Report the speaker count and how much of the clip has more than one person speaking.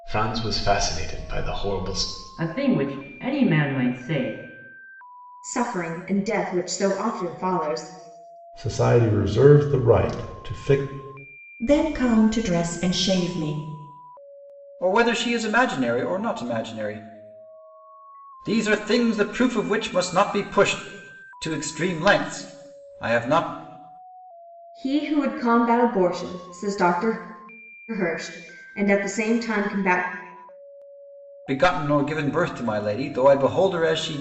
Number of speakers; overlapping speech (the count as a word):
six, no overlap